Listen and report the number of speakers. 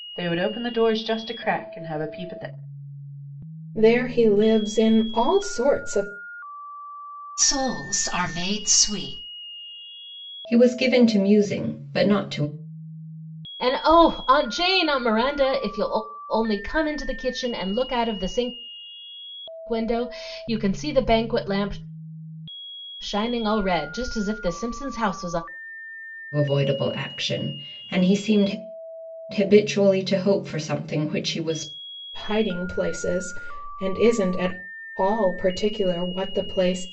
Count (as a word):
five